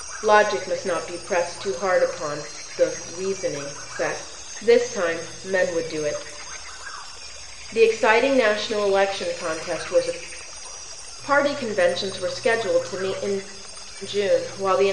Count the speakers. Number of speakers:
1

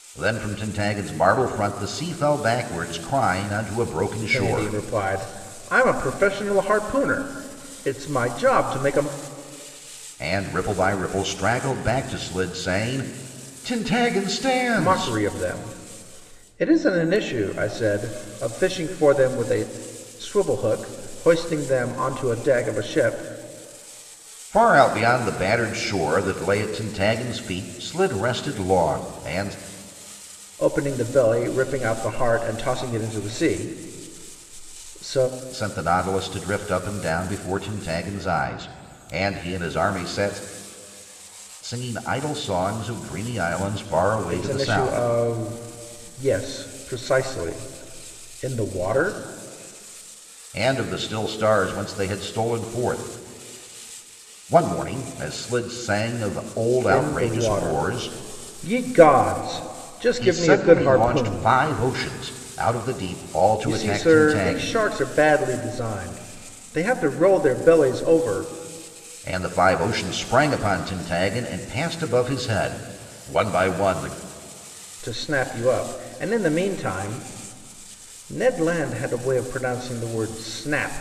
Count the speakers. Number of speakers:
2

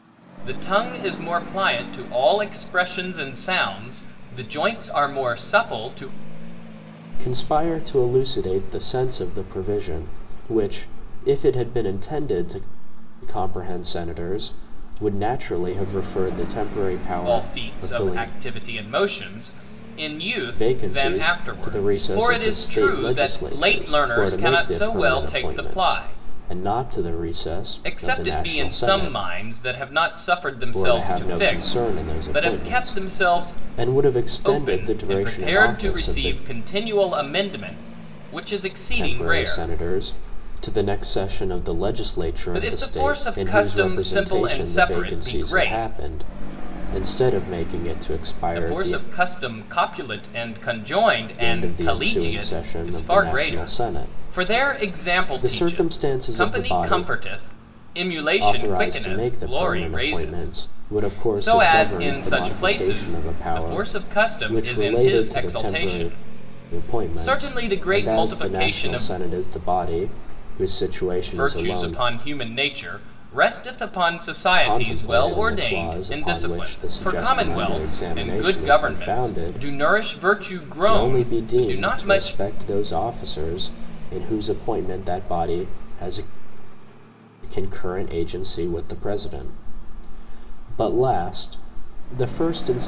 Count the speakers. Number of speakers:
2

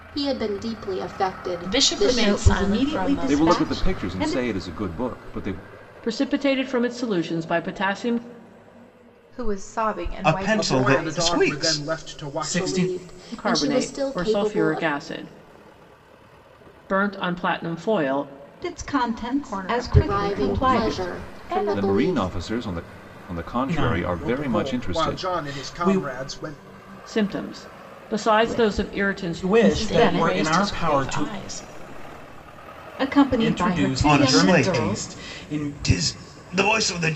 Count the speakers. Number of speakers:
9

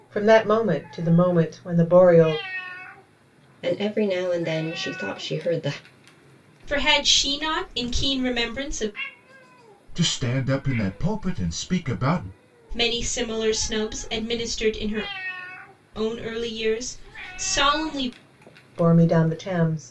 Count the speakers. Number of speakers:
4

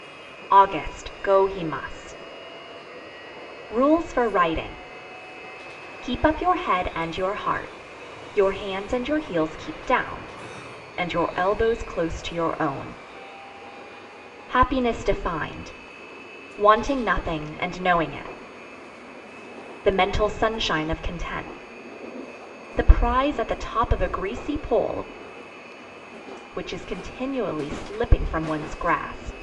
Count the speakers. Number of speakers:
1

